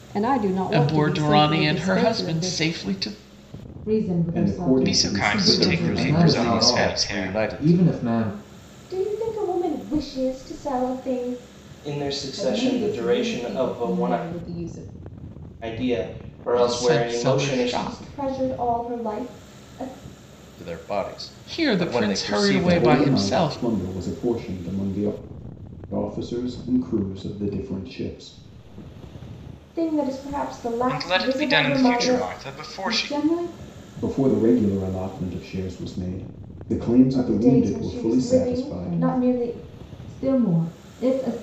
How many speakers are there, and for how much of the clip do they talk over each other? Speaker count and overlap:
ten, about 38%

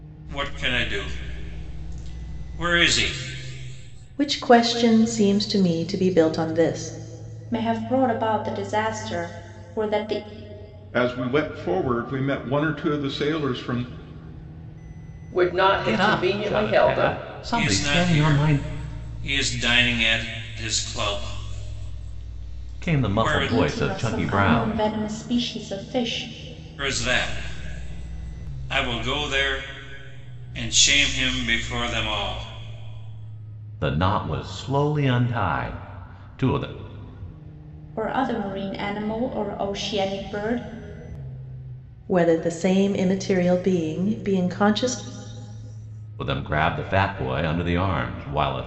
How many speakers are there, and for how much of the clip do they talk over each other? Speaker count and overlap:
six, about 10%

